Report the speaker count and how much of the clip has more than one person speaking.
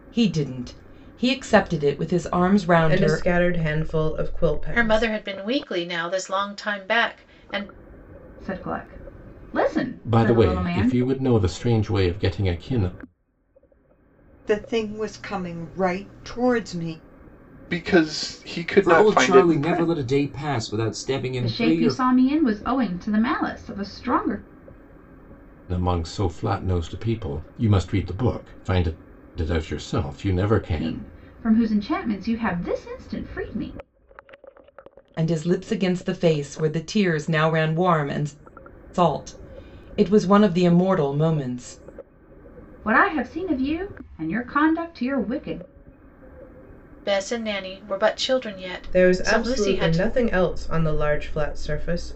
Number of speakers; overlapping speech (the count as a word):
eight, about 10%